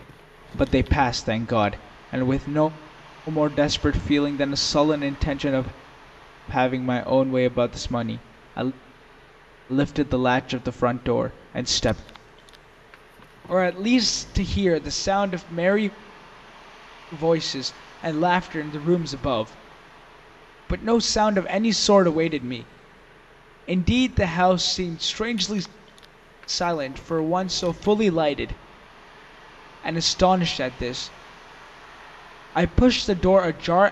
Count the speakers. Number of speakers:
one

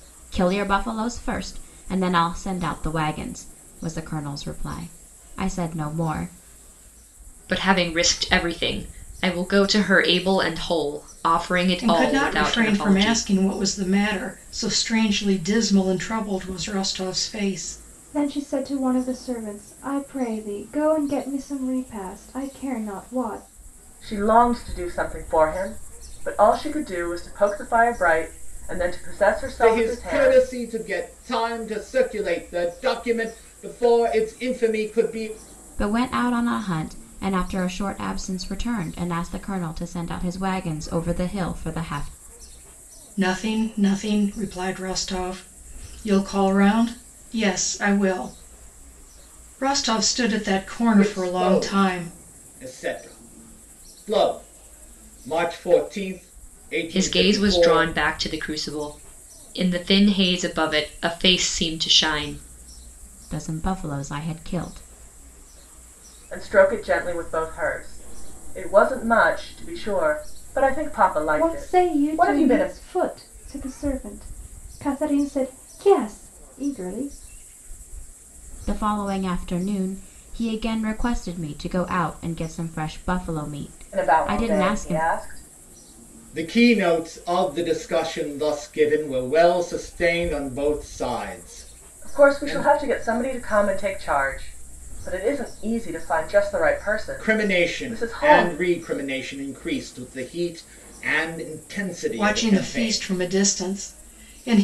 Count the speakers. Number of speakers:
six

